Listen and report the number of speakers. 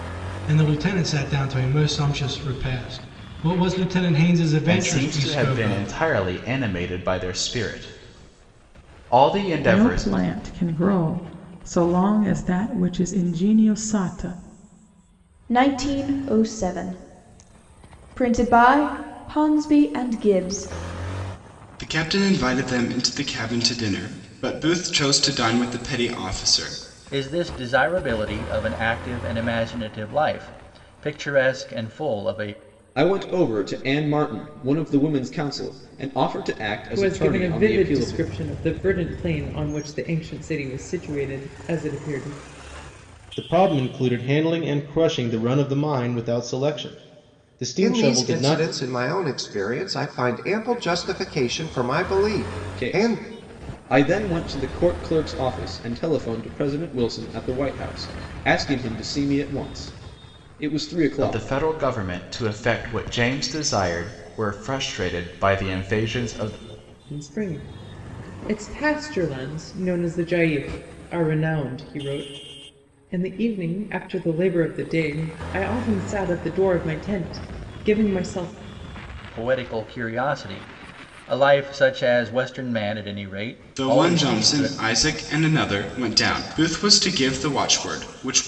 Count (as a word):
ten